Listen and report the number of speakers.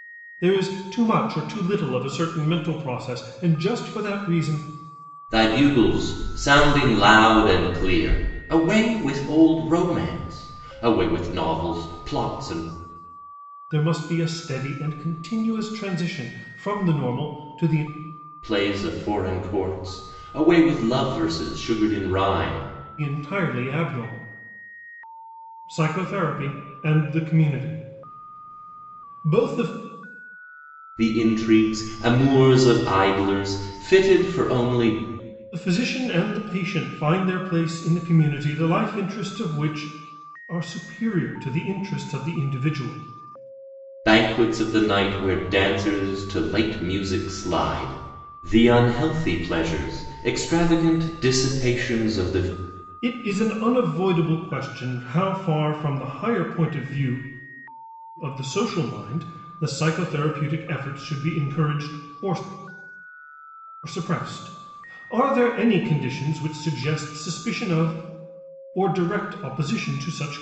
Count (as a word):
two